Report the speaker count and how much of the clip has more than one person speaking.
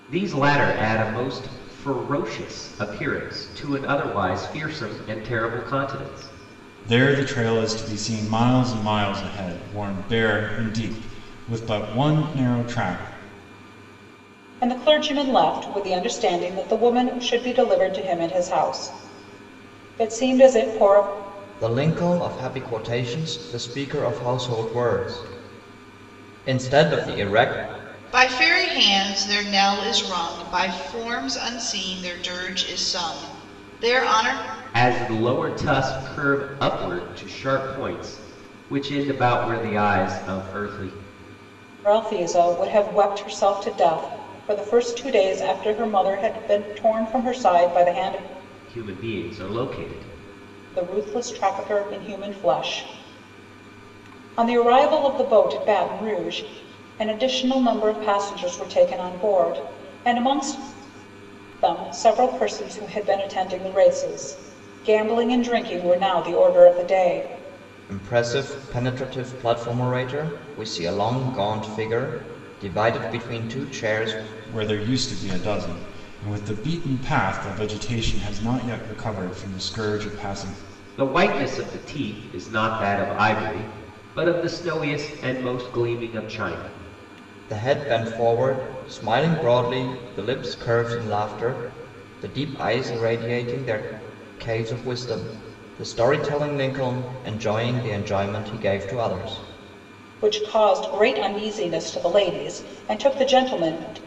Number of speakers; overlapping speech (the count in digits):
5, no overlap